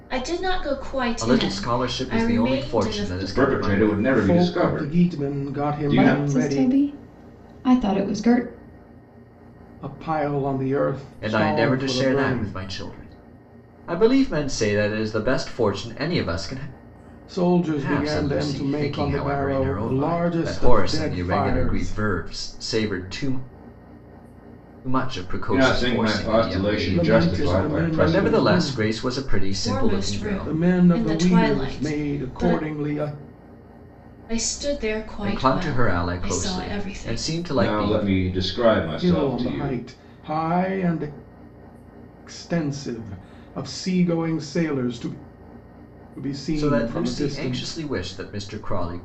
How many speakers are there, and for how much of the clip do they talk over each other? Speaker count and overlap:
5, about 46%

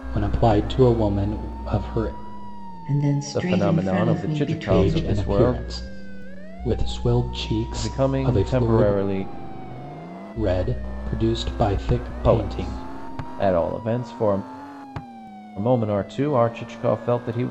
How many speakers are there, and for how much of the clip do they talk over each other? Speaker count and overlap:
3, about 25%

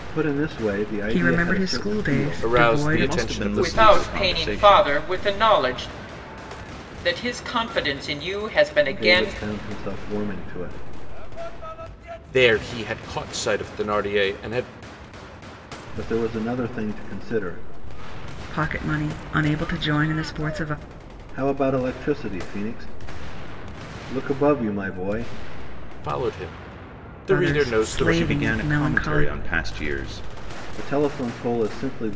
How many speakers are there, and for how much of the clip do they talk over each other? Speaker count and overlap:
5, about 20%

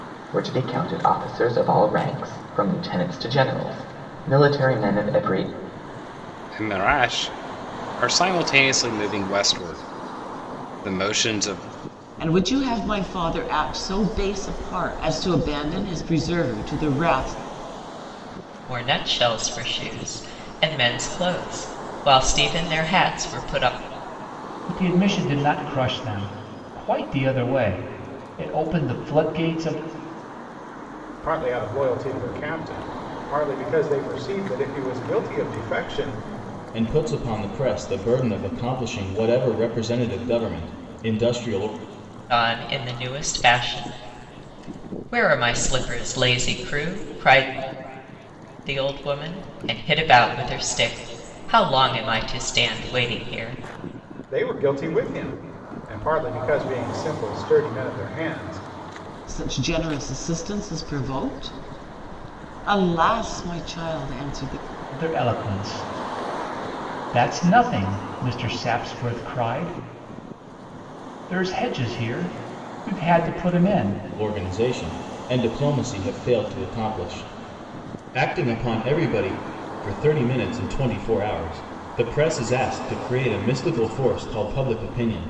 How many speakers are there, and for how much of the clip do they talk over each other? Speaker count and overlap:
7, no overlap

